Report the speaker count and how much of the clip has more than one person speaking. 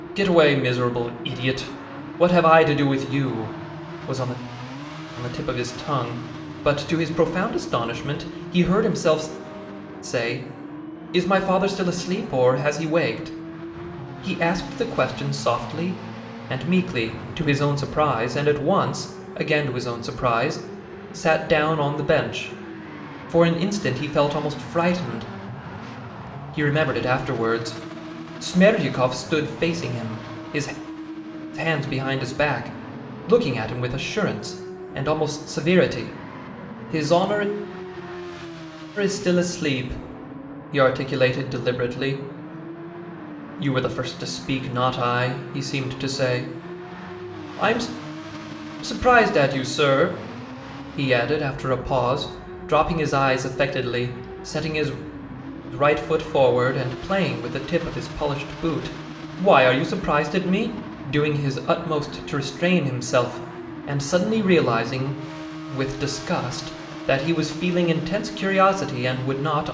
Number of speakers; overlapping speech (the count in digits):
1, no overlap